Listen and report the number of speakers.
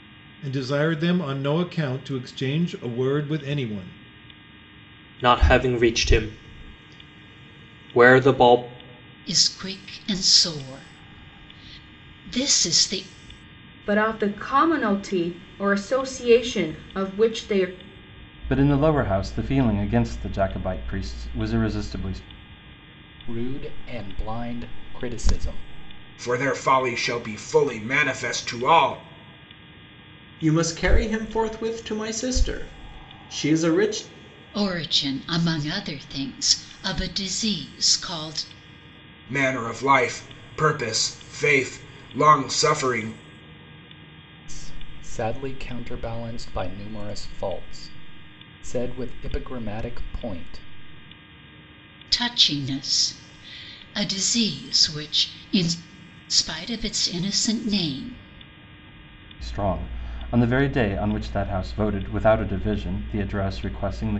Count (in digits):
8